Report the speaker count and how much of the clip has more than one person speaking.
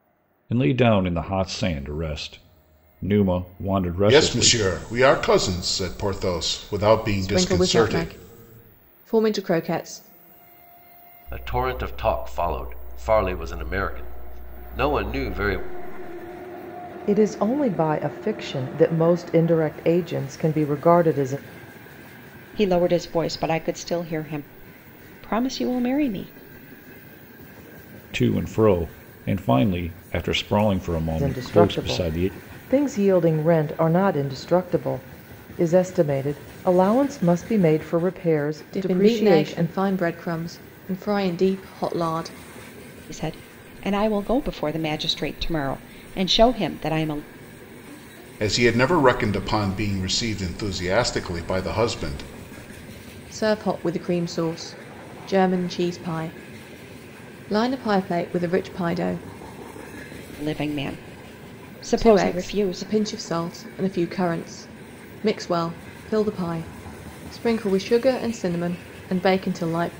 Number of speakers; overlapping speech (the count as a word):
six, about 7%